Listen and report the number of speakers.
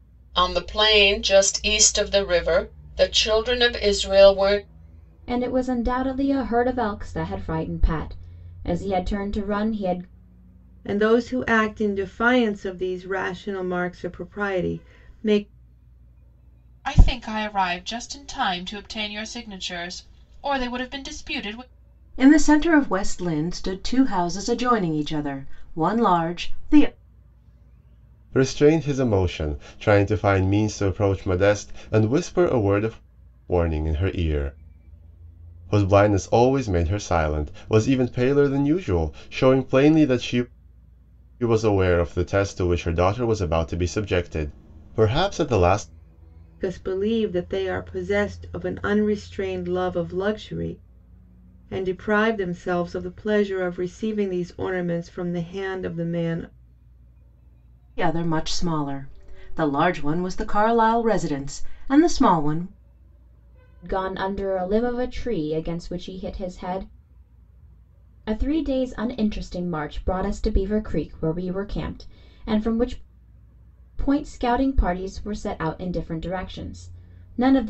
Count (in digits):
6